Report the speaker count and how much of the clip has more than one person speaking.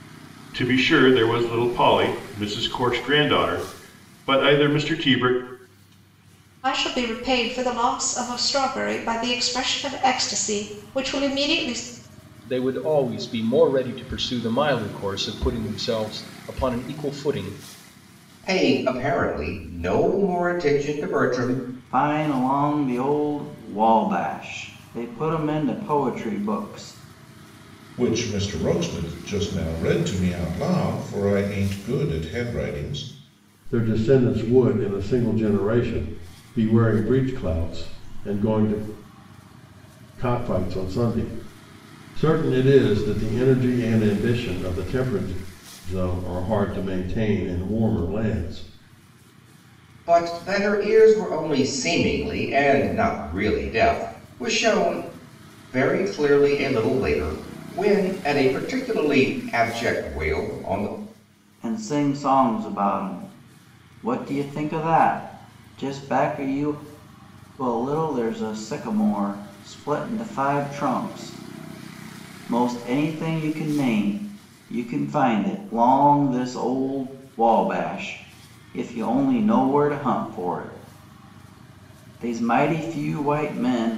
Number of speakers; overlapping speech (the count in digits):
7, no overlap